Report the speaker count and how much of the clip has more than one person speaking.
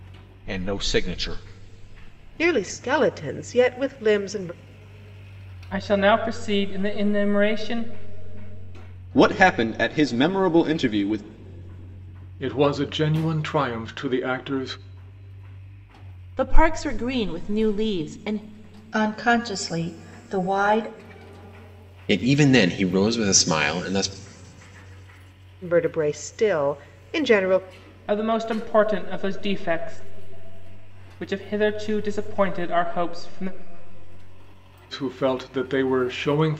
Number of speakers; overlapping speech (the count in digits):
8, no overlap